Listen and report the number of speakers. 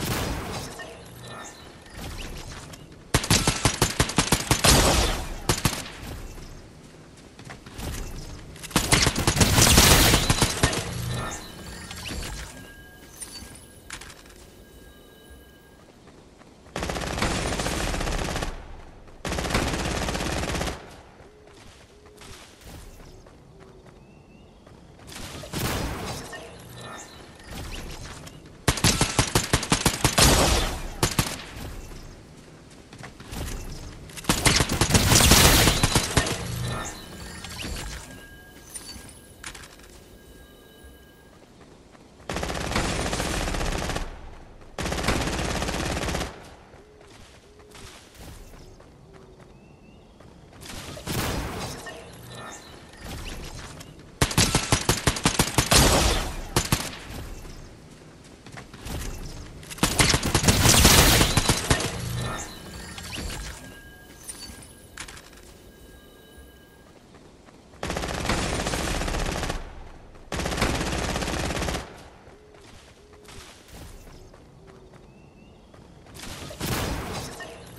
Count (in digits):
0